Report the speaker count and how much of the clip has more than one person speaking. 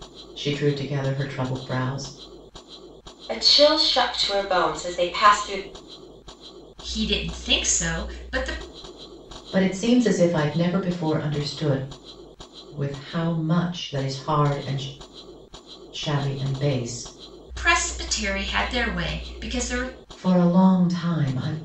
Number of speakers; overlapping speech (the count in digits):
3, no overlap